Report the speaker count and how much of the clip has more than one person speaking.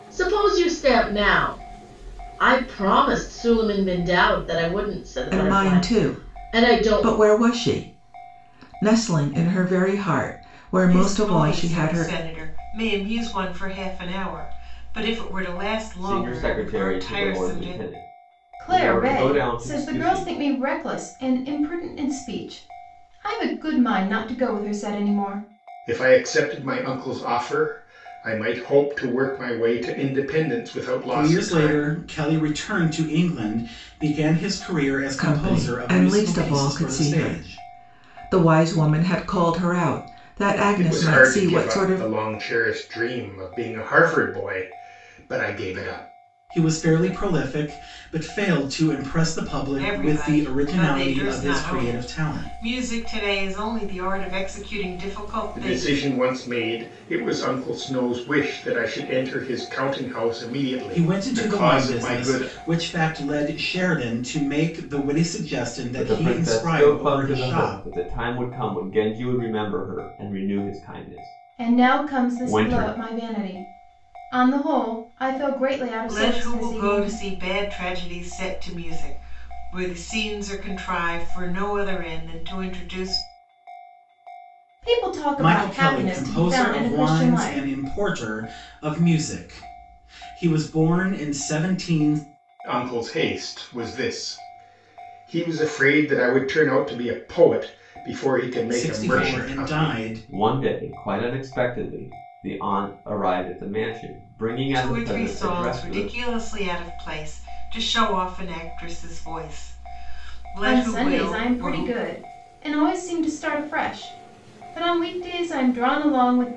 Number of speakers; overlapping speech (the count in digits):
7, about 24%